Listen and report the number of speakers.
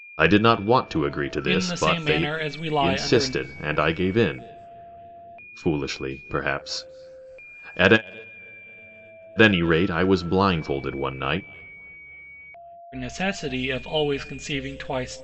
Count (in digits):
2